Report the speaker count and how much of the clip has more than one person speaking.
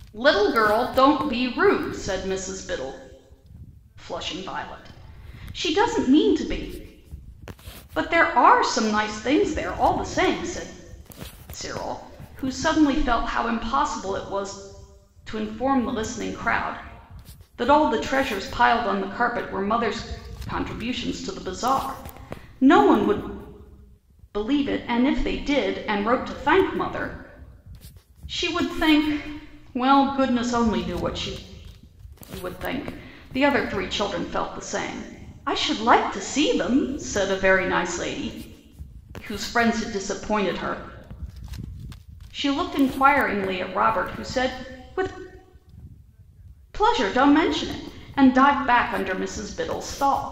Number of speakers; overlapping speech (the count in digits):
1, no overlap